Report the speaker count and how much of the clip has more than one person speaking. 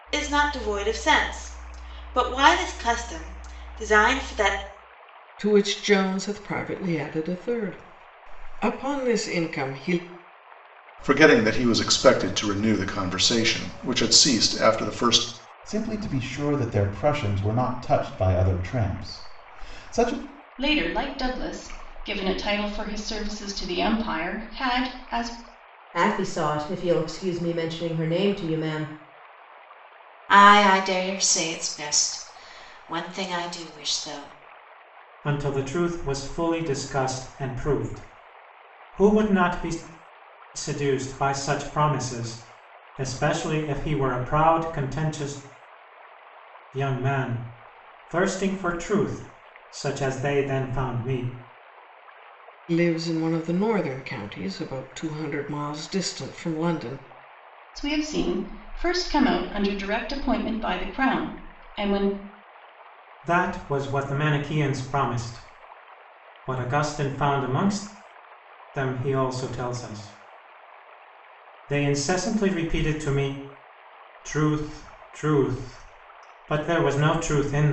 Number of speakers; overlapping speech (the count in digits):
8, no overlap